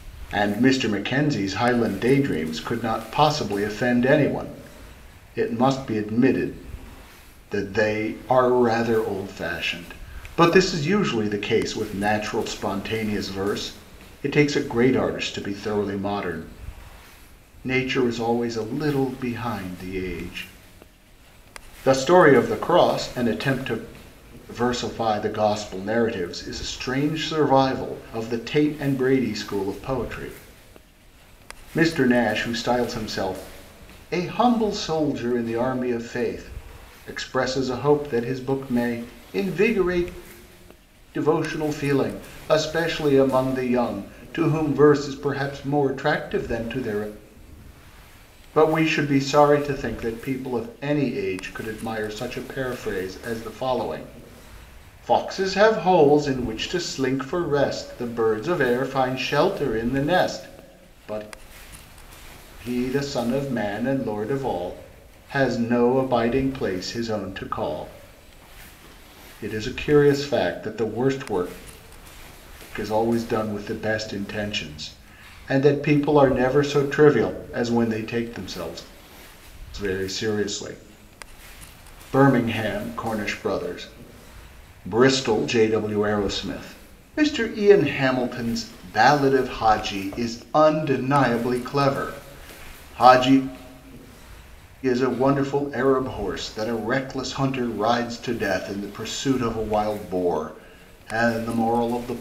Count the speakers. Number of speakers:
1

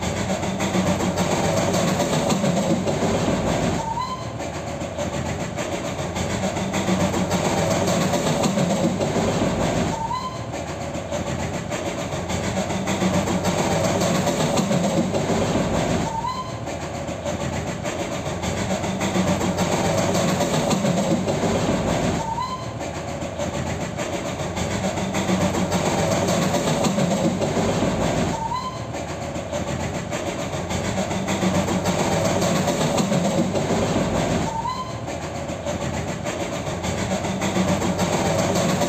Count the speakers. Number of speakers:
0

